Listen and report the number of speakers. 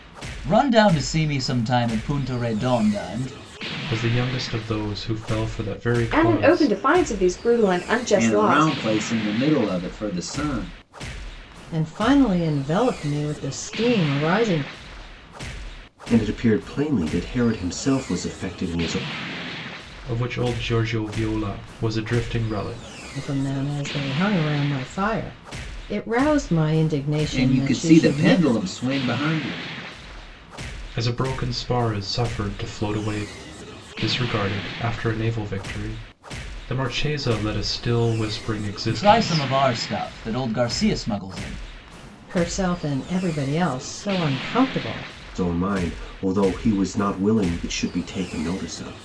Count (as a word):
six